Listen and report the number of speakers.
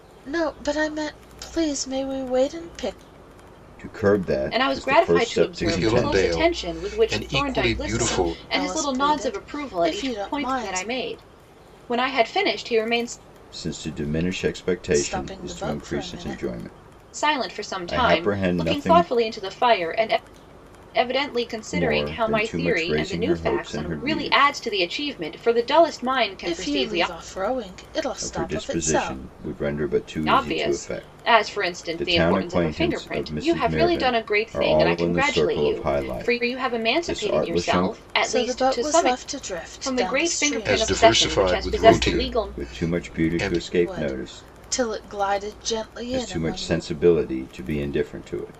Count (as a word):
four